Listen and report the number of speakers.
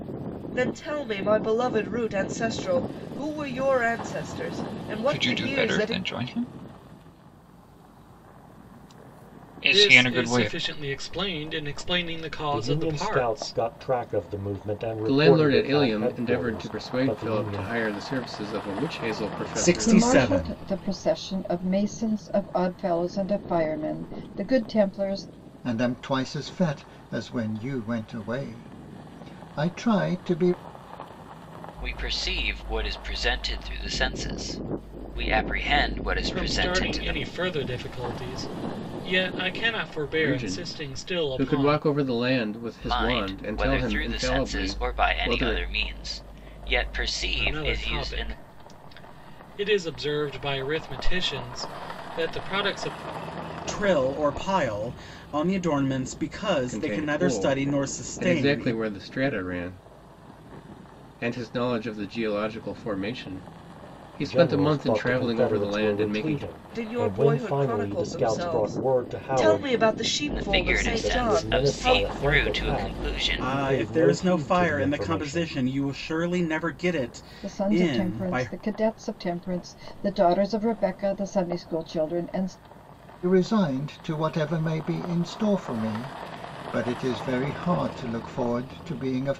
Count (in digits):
9